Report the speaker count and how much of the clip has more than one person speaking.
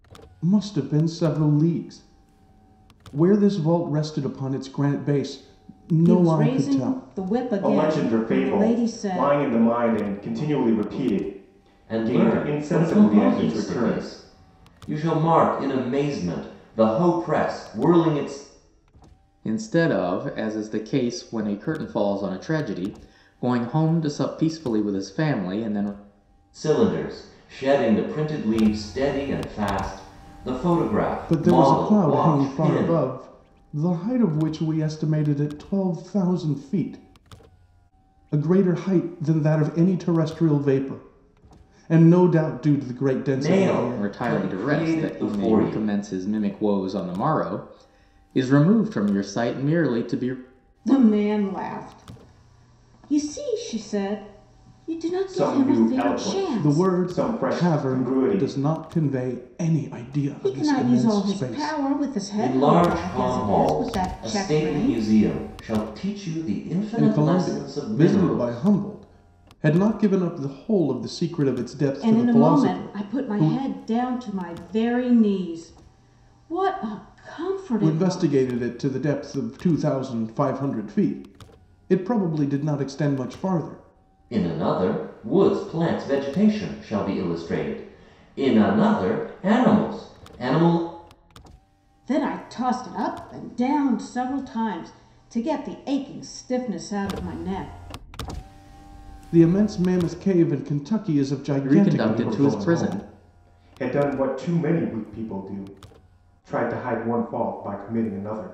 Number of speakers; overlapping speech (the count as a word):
five, about 20%